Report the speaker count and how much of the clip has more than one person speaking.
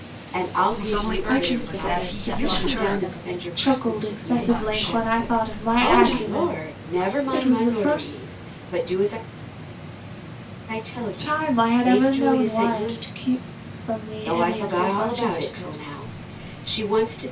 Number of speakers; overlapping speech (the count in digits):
3, about 63%